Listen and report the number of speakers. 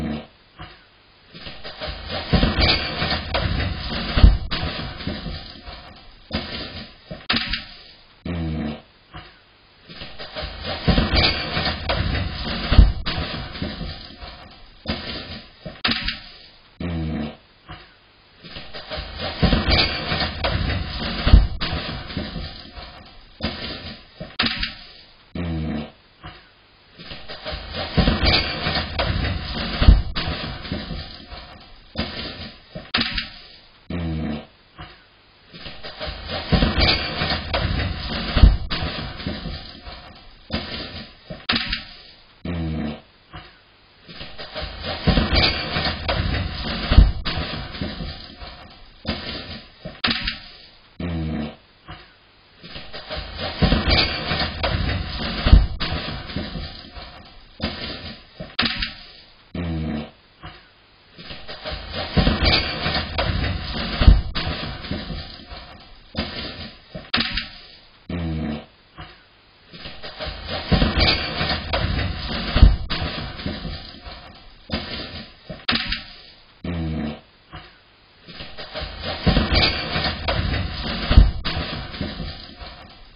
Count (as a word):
zero